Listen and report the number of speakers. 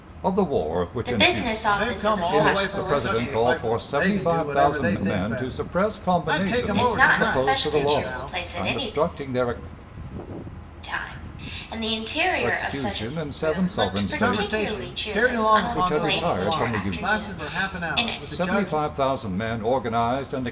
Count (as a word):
three